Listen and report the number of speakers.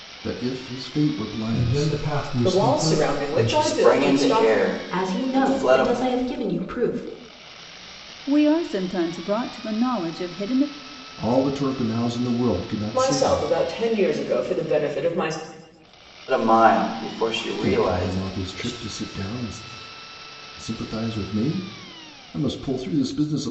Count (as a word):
six